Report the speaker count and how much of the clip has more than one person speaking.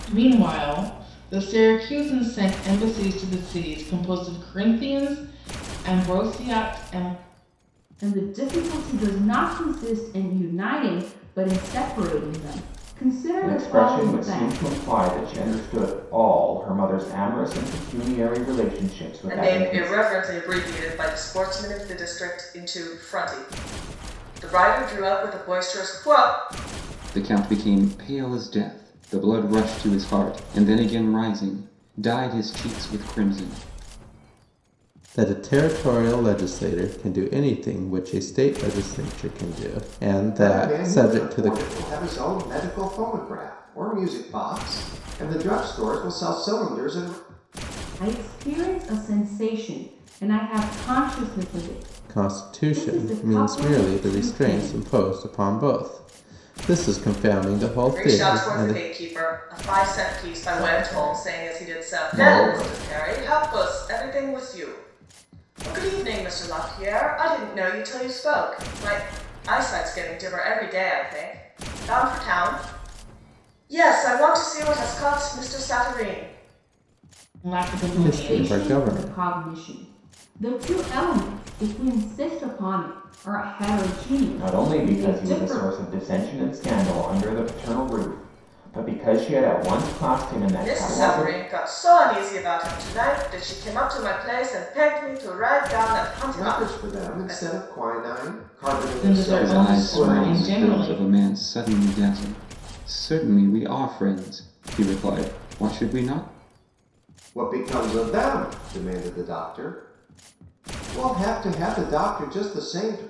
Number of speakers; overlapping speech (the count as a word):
seven, about 14%